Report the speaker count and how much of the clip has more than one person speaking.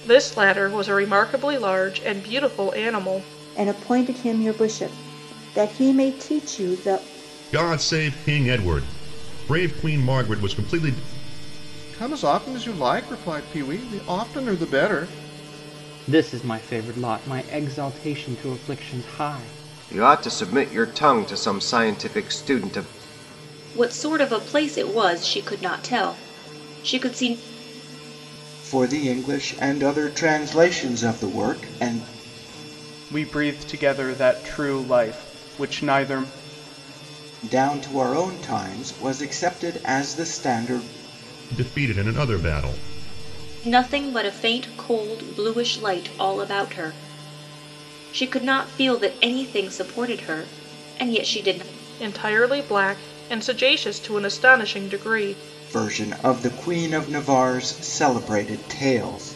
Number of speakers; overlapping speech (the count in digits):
9, no overlap